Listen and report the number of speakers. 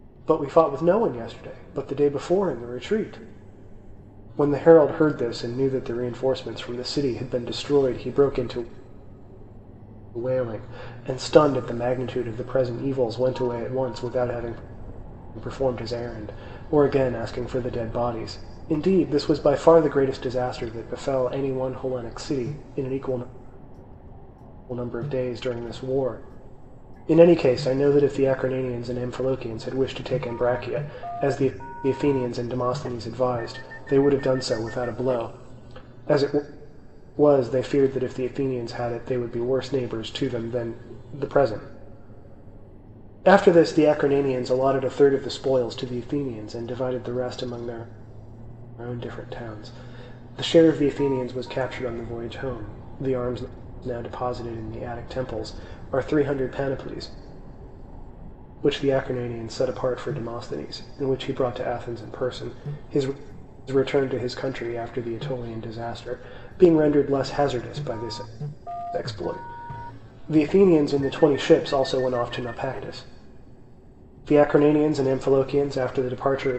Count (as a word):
one